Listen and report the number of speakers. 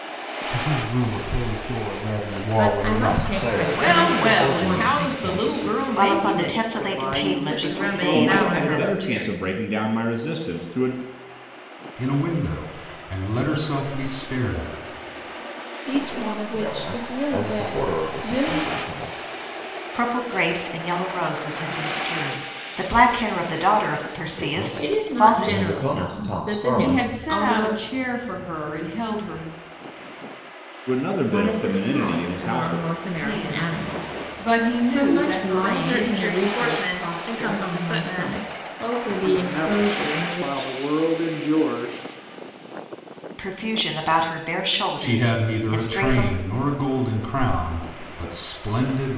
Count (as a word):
ten